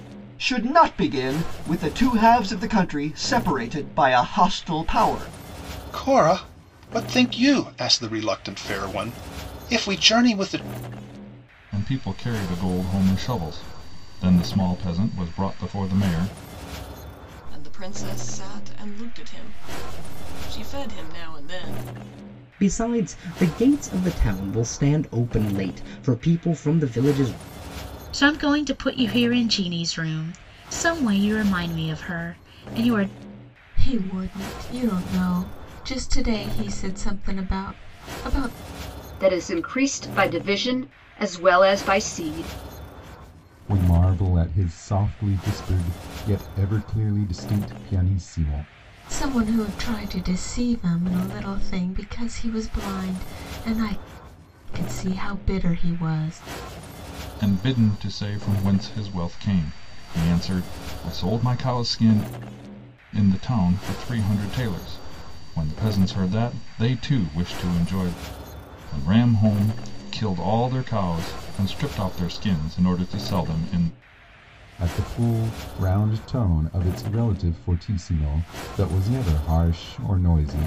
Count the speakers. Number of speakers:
9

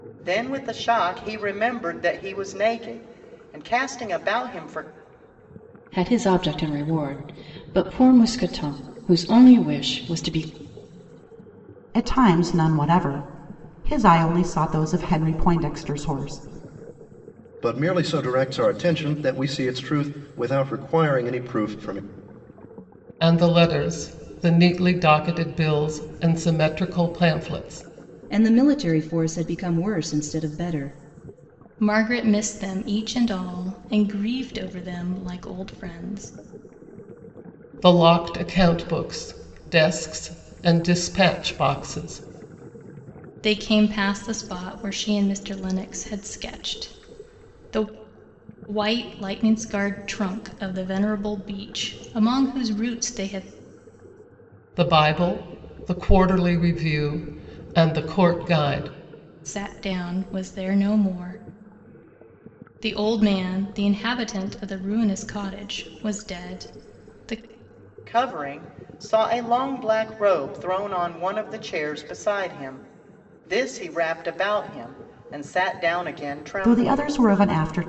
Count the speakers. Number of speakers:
7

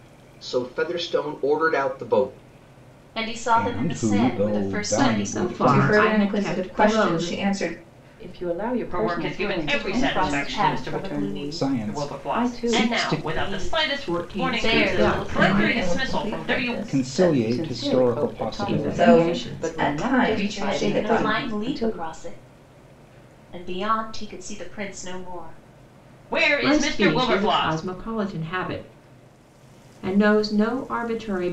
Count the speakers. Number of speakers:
7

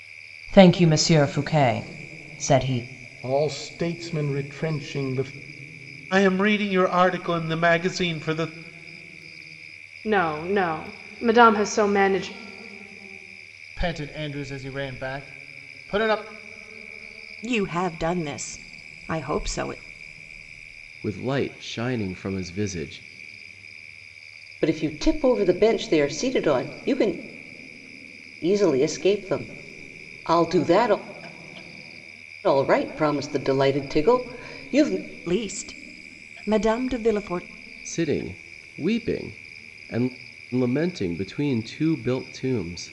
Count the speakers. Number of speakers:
8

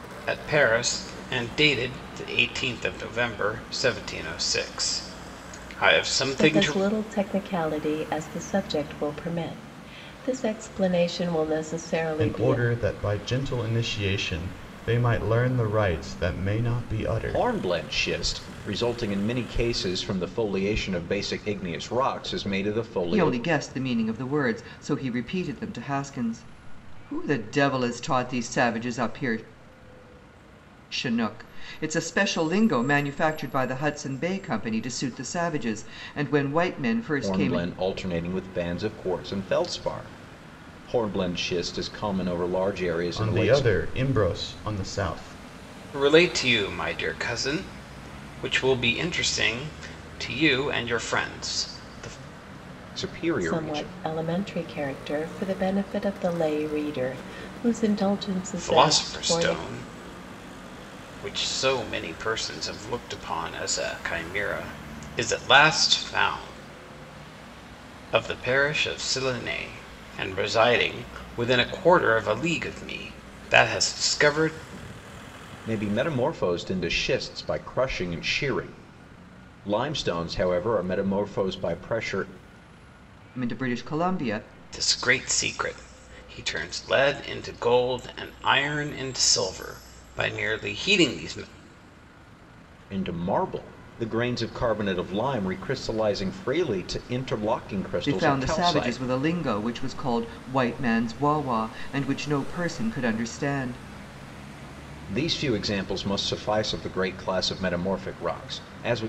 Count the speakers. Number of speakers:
5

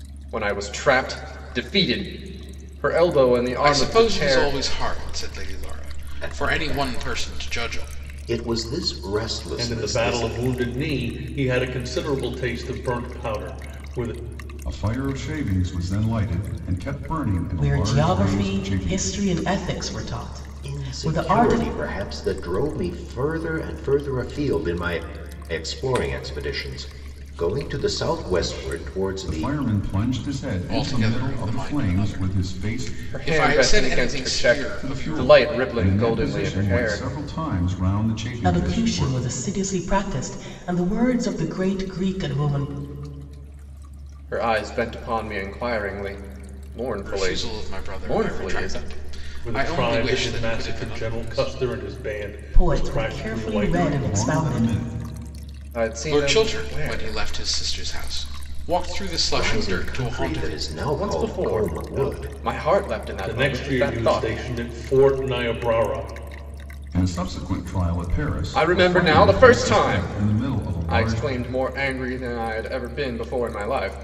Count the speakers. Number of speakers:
6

